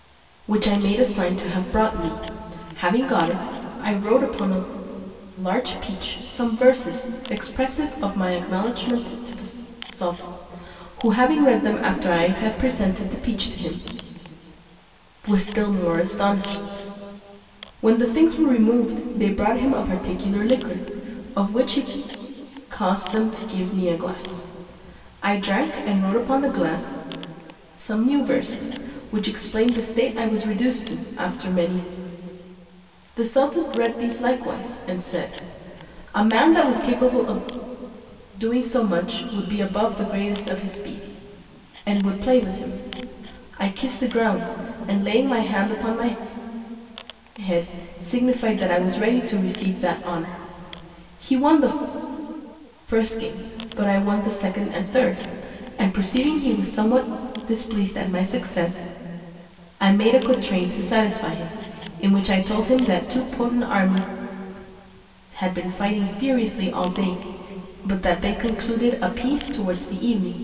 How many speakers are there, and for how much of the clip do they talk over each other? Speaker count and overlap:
one, no overlap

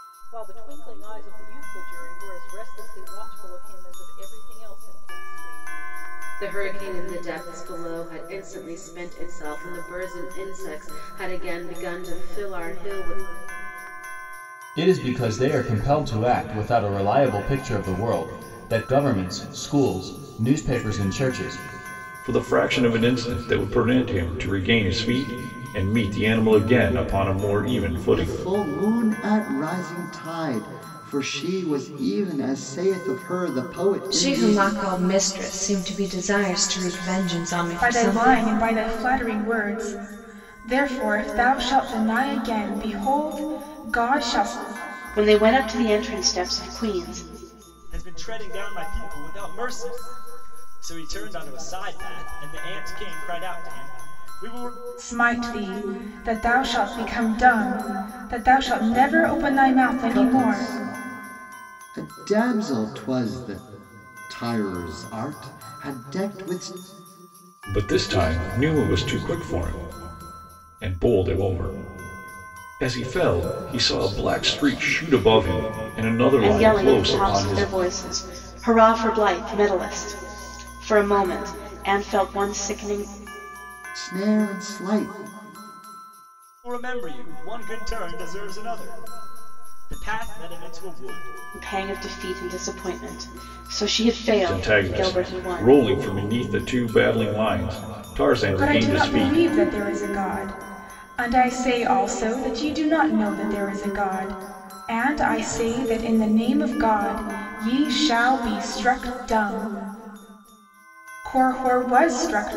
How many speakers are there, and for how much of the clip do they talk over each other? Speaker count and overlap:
nine, about 6%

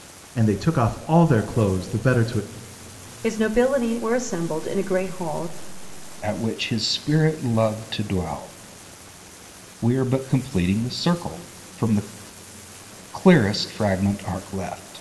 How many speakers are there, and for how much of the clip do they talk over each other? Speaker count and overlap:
three, no overlap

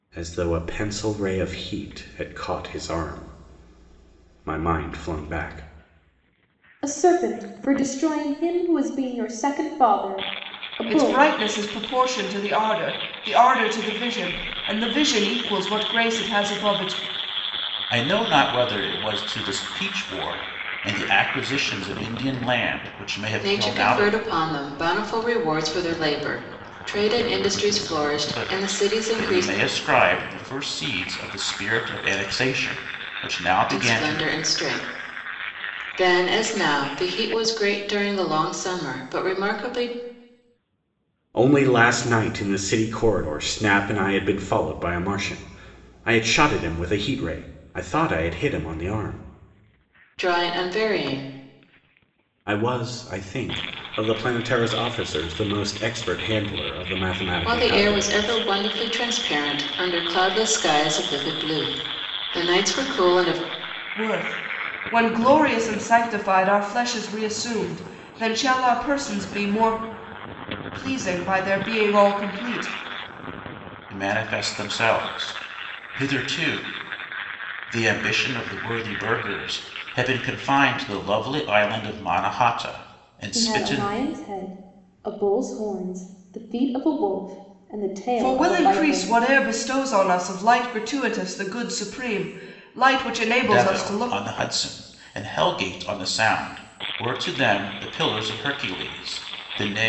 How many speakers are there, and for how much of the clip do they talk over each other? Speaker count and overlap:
five, about 6%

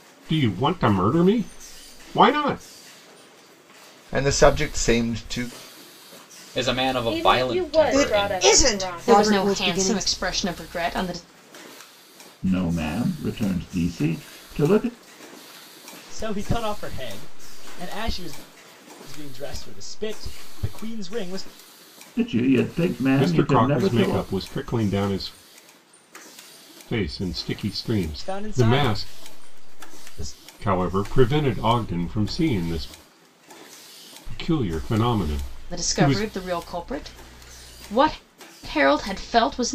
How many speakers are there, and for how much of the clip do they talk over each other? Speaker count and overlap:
eight, about 14%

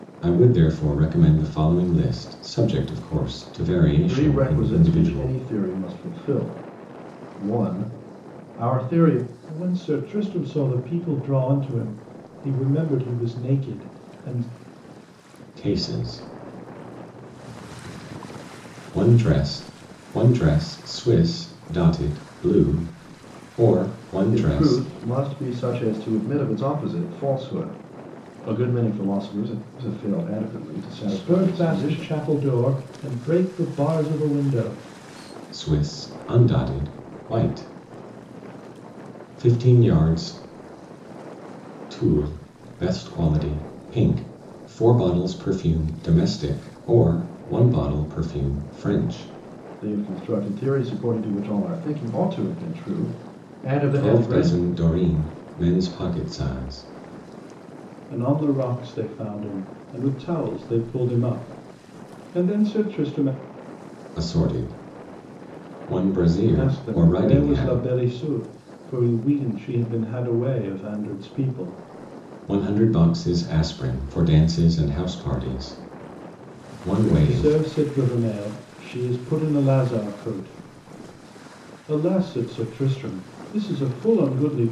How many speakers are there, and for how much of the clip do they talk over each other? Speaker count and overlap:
three, about 6%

